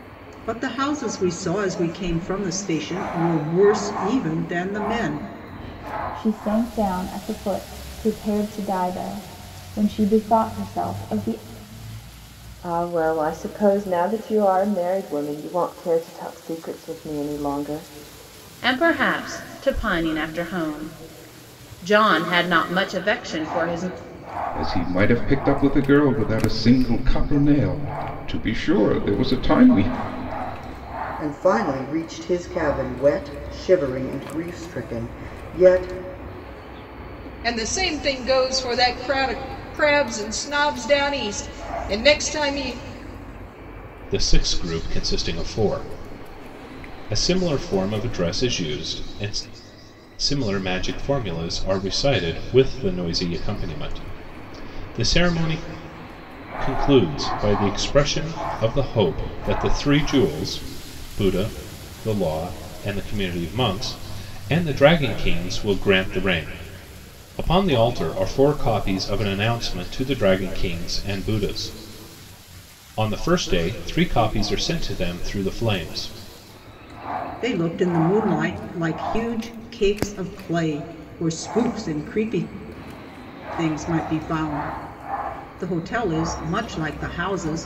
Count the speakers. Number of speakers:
eight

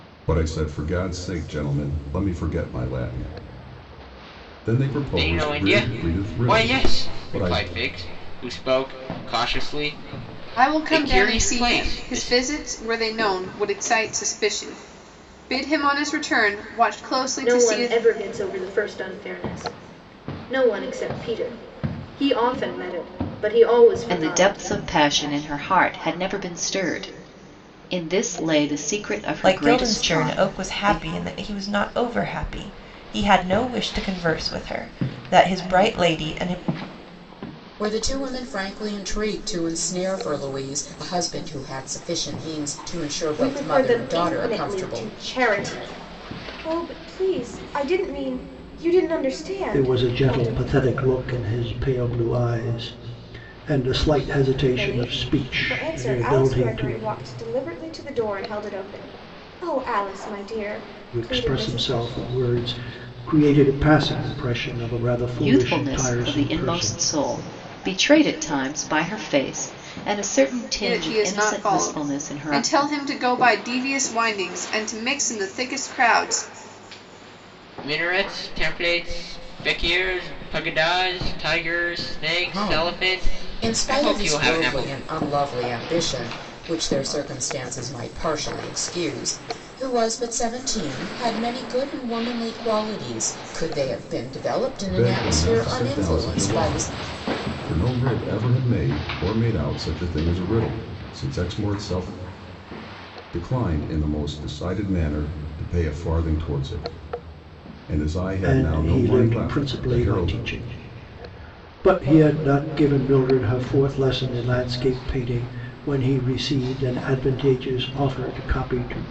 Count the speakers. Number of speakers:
nine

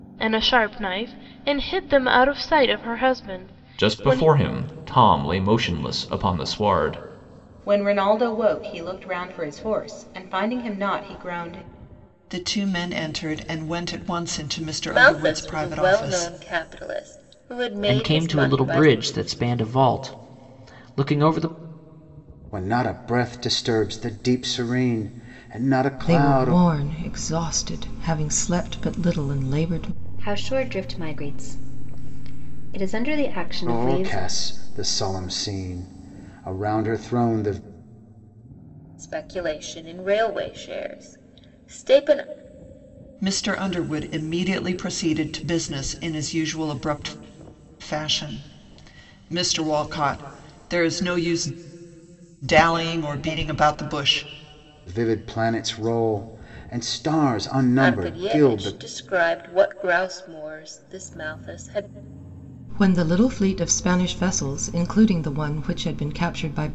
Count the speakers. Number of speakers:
nine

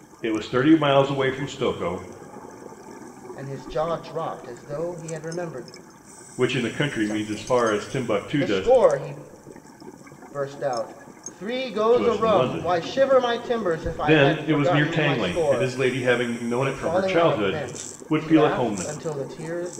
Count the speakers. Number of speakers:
two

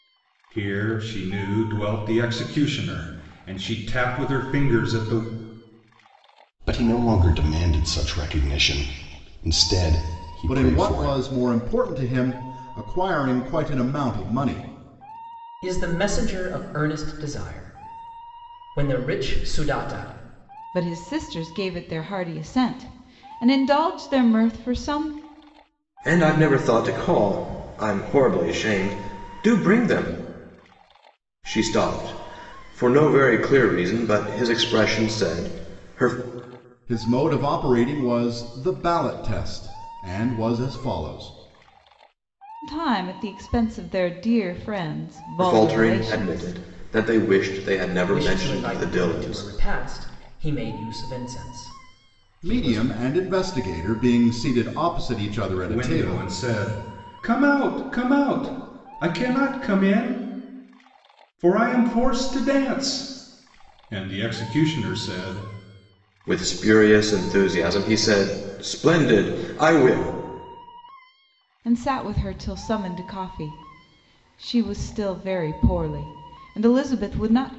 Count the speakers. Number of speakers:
six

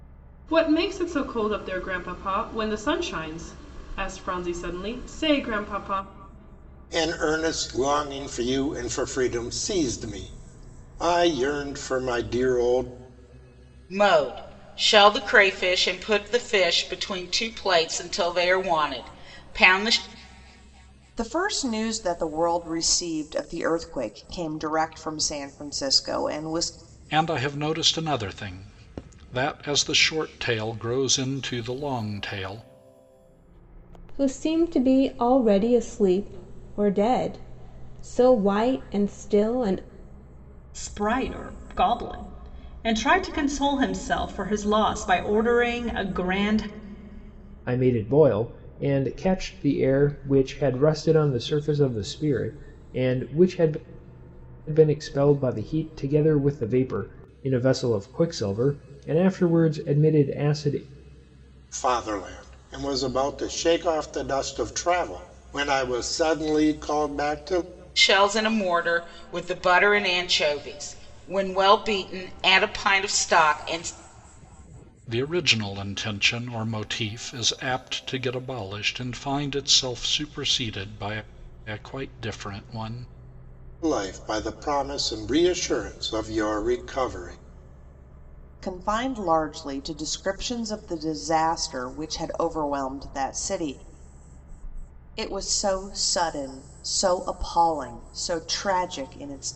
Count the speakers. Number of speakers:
eight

